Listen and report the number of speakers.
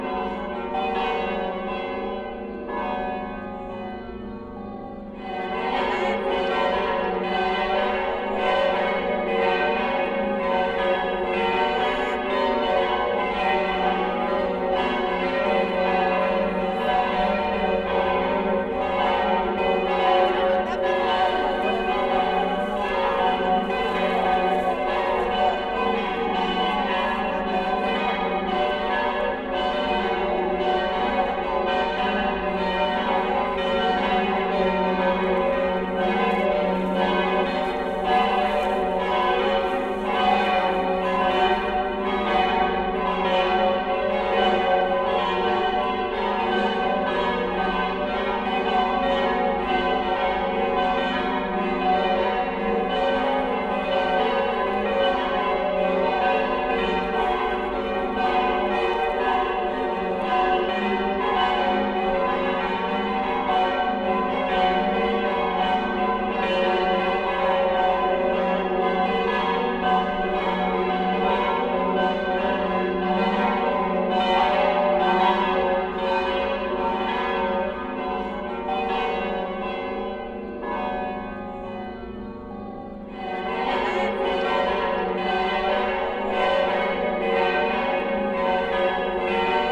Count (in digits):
0